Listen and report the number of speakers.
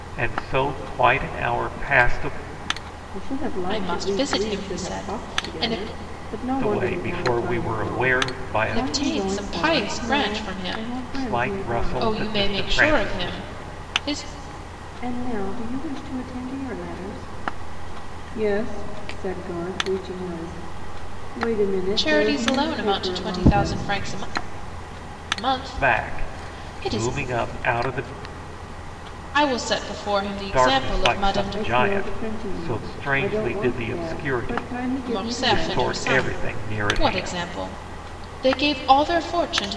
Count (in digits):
3